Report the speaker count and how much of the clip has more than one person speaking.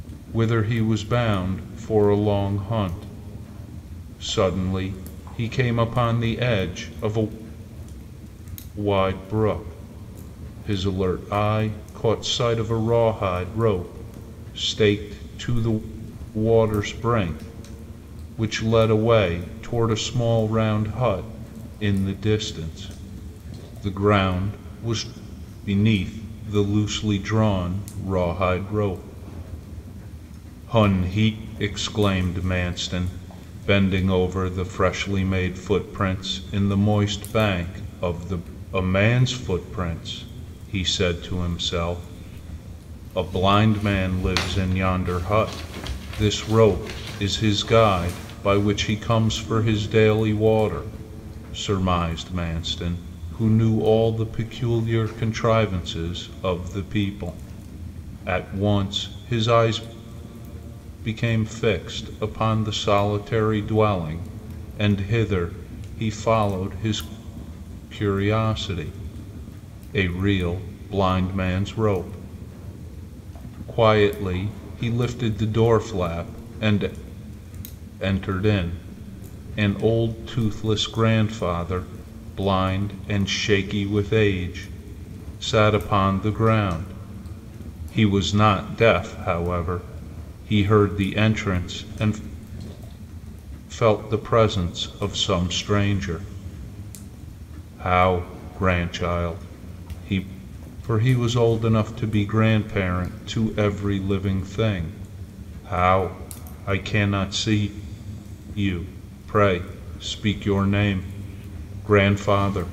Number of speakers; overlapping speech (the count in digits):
1, no overlap